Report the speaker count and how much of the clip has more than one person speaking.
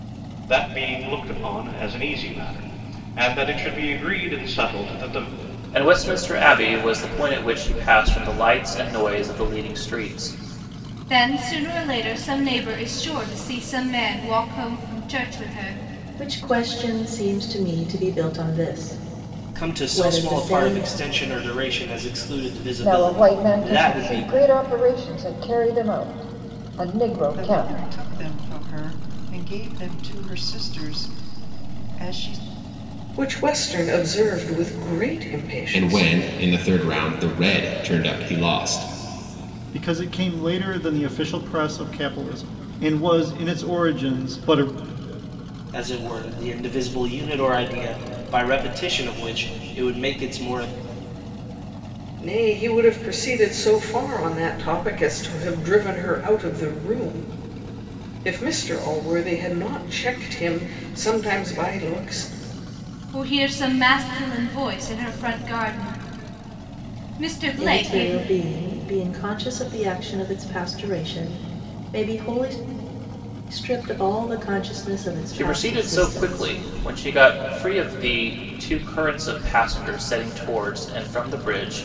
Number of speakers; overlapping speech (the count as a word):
ten, about 7%